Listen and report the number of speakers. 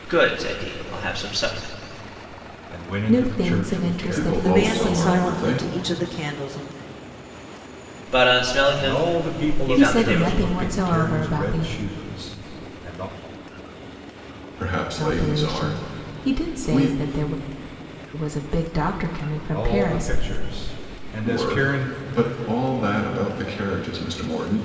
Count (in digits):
5